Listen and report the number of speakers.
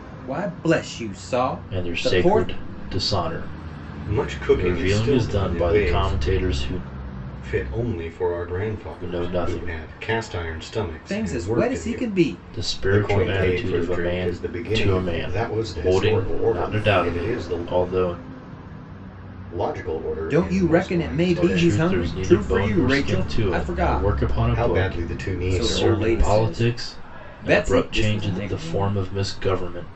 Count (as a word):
three